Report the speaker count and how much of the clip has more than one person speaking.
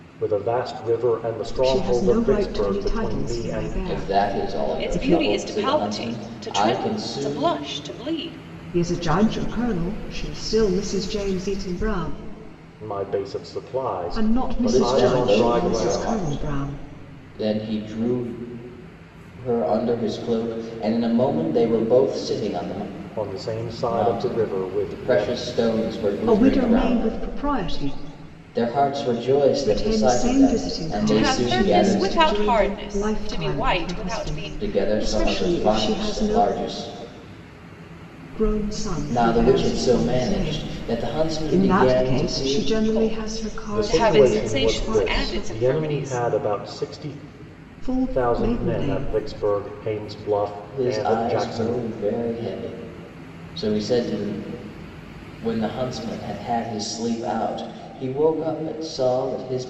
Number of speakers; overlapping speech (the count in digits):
4, about 46%